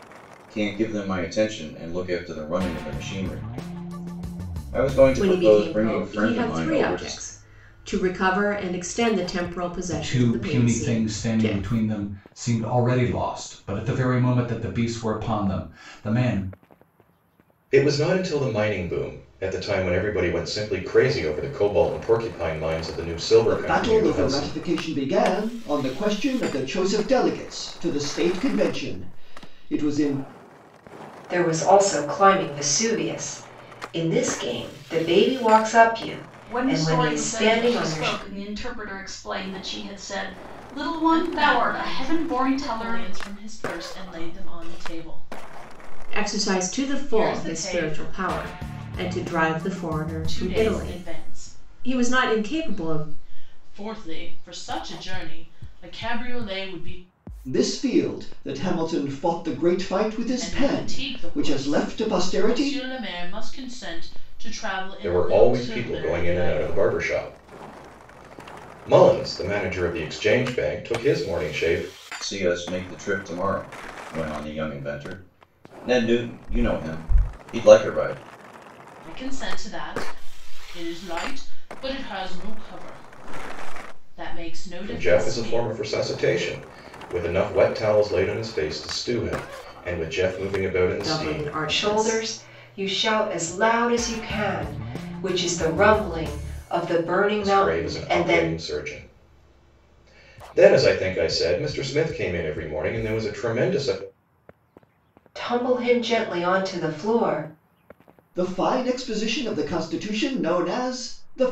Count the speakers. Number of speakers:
8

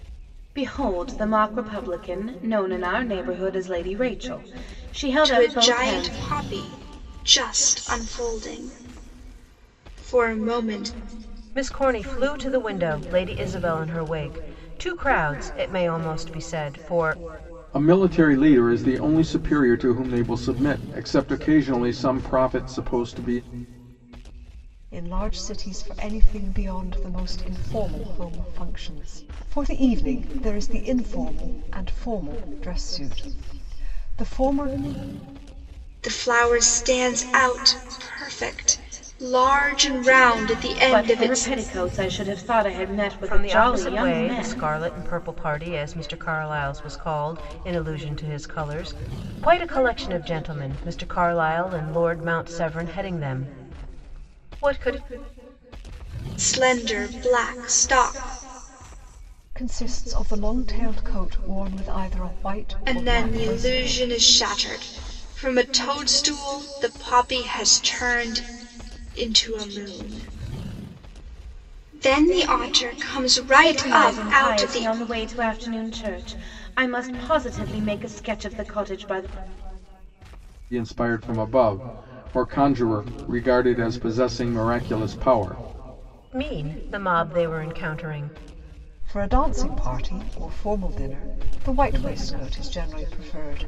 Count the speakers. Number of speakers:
5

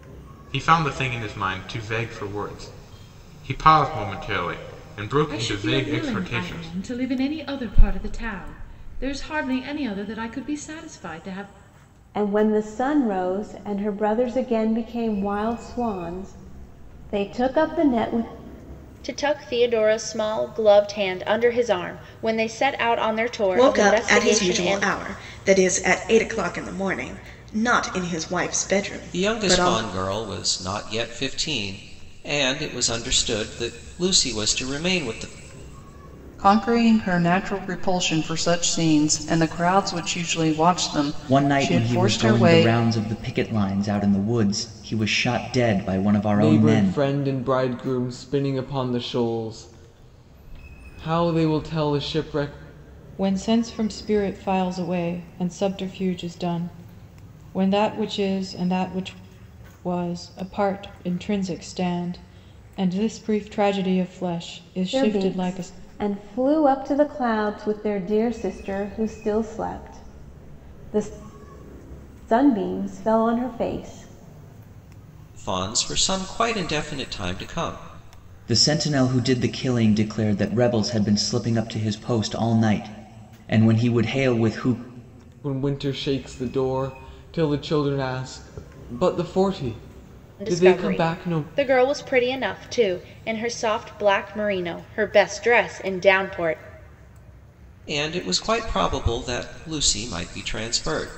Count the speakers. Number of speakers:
10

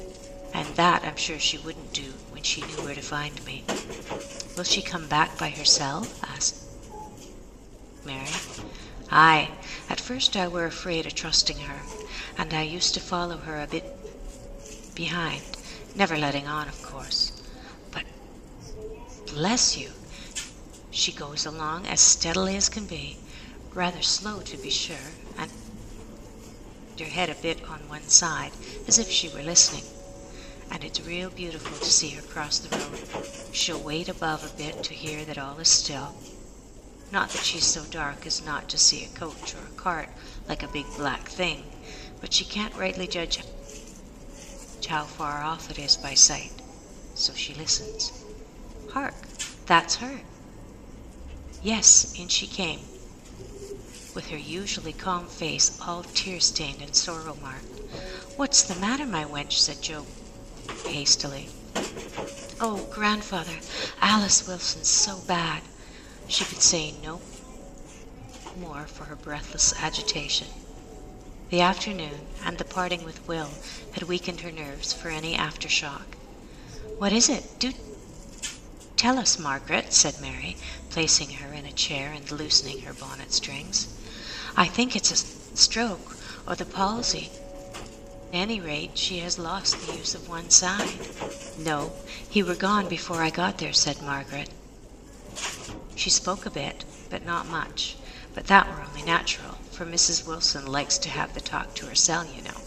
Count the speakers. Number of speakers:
1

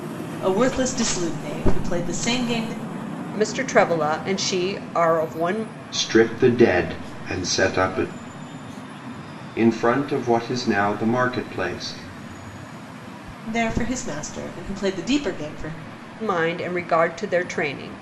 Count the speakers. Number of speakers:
3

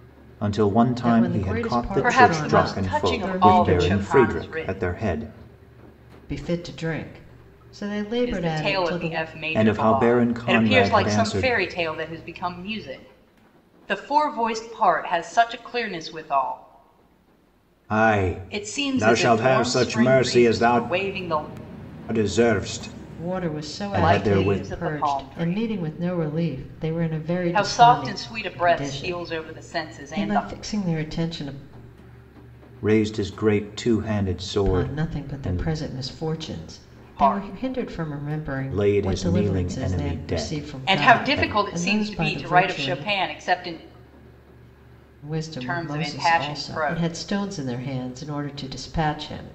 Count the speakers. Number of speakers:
3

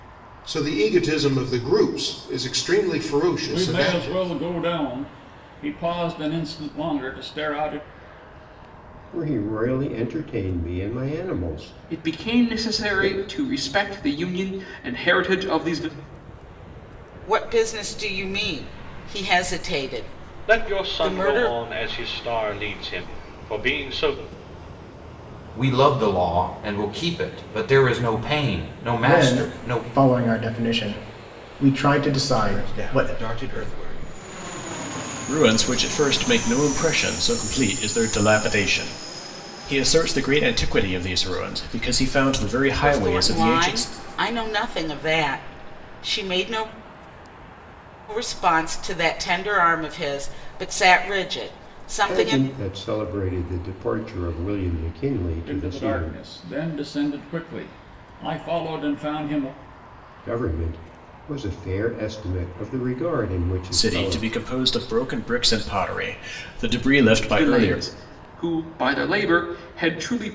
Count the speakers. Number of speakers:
10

